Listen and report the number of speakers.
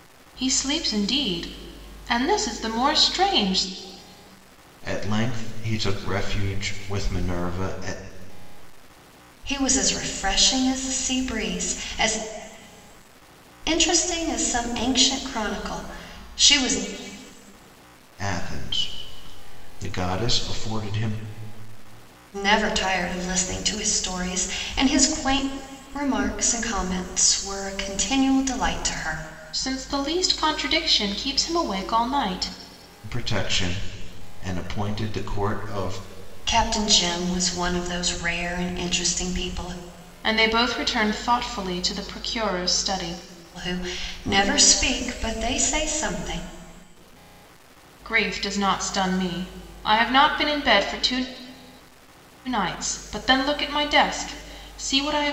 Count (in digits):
3